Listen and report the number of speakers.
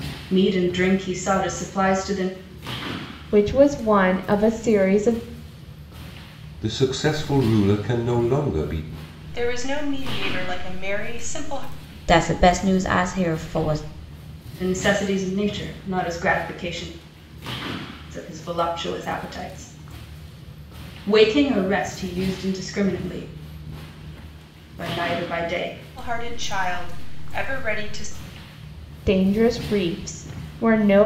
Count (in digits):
5